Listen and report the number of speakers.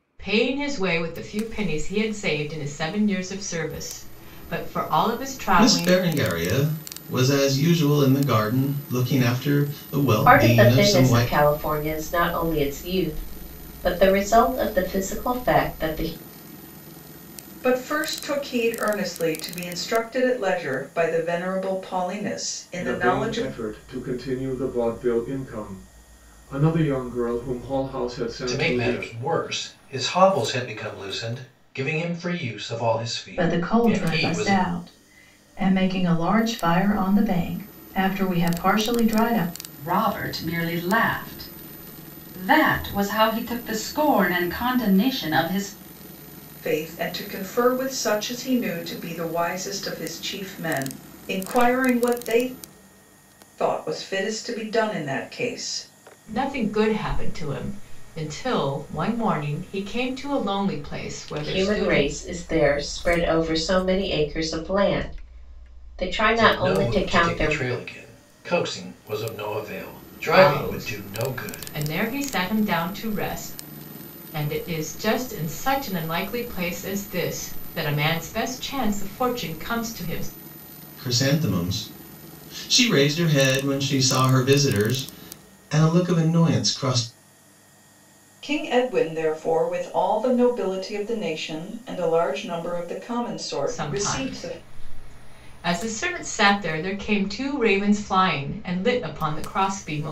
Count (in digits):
8